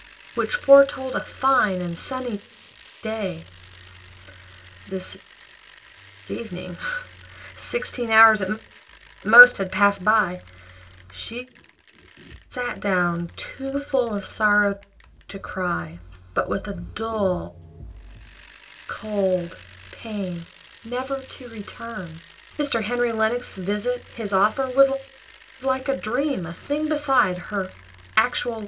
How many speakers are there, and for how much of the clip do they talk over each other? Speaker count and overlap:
1, no overlap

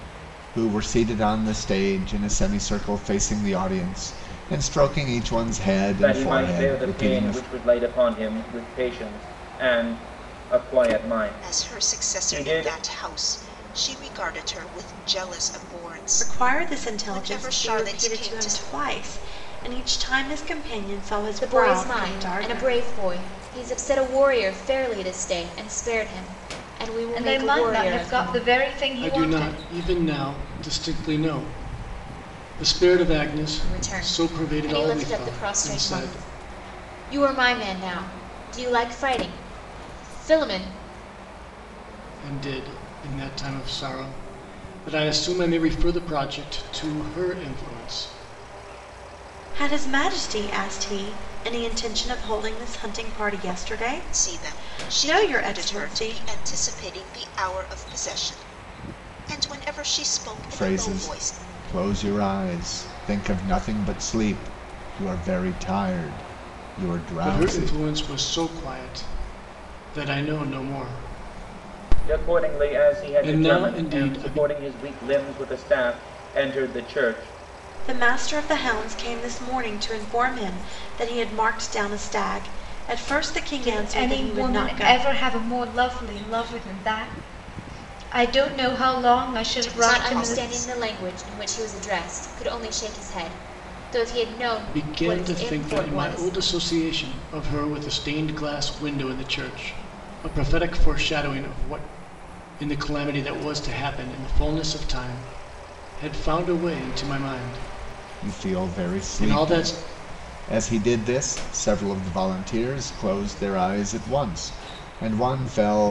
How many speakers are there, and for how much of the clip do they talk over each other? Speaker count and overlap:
7, about 20%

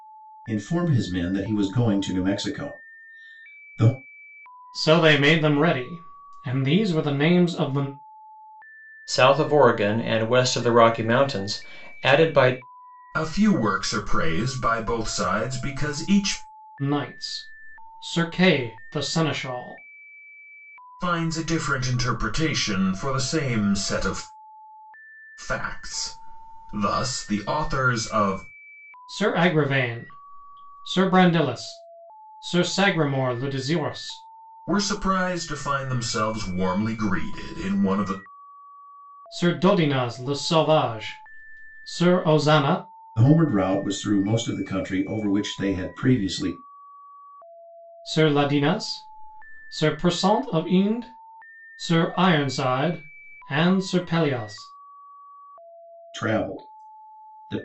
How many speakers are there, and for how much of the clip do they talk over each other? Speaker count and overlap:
4, no overlap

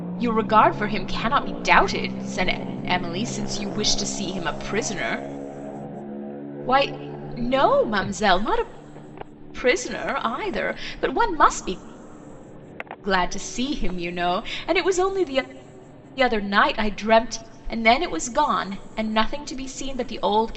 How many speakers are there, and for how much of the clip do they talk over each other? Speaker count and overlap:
1, no overlap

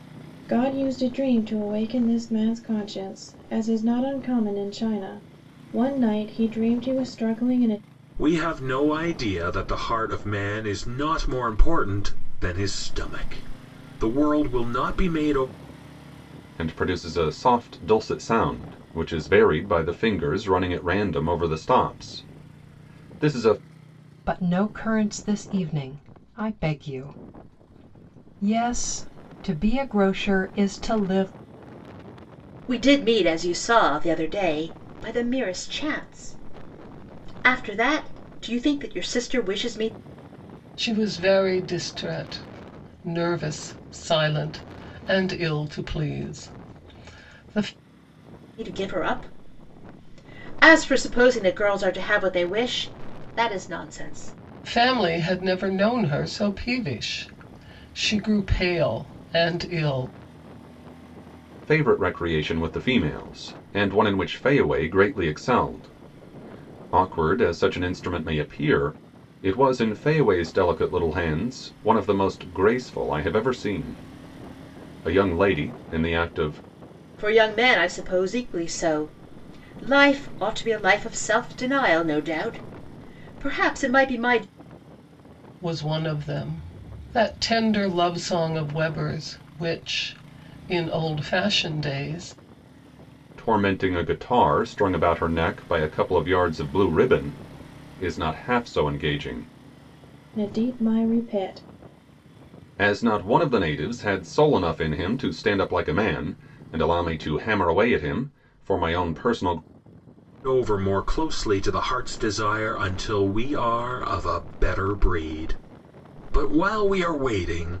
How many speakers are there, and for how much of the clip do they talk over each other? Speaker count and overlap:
6, no overlap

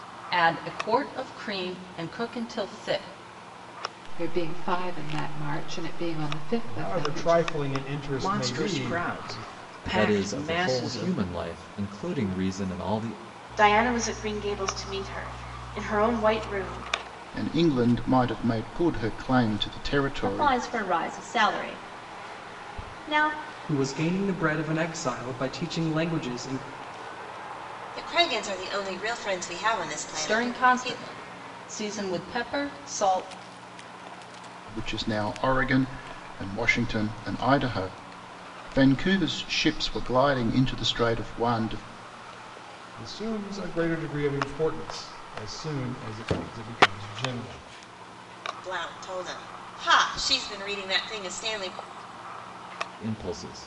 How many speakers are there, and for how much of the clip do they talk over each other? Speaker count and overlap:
10, about 9%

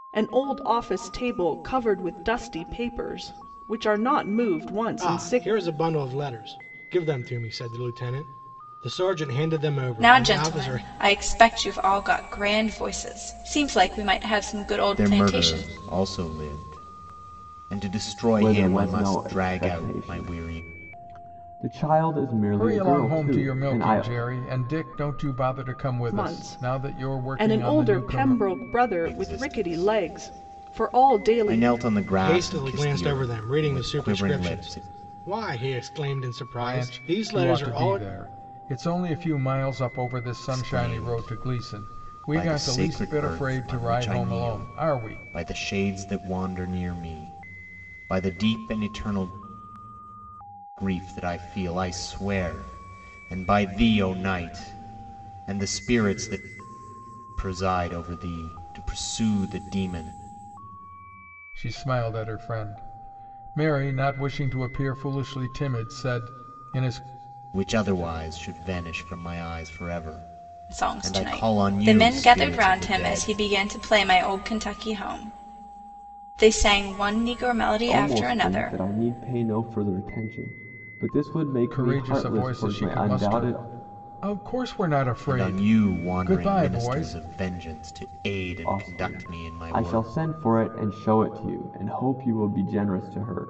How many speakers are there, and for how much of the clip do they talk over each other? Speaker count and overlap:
6, about 31%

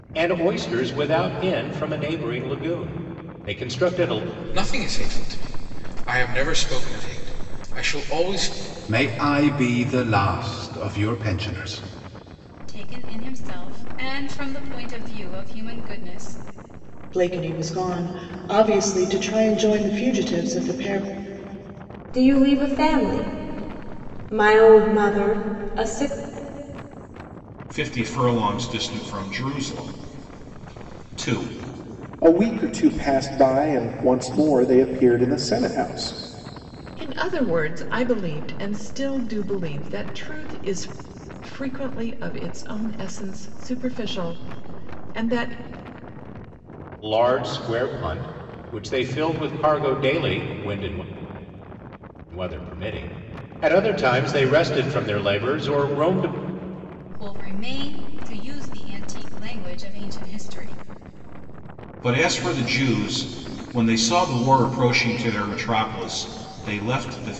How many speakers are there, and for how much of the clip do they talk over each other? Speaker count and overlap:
9, no overlap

